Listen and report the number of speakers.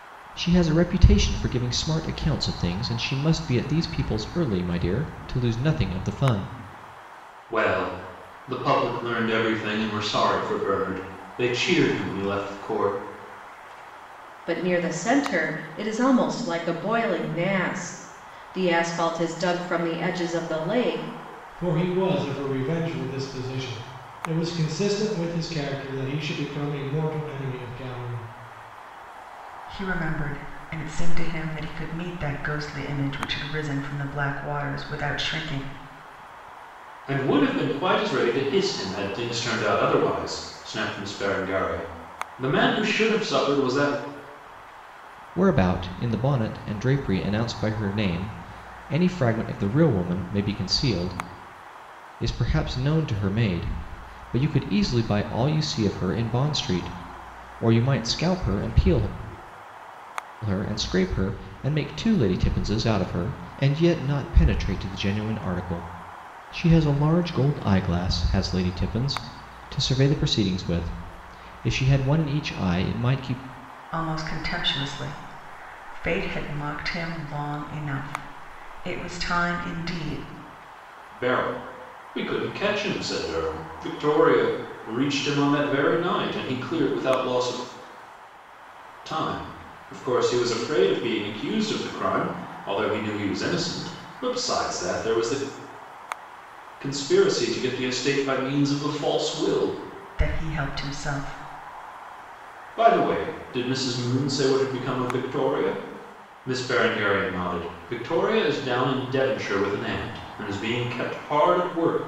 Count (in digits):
5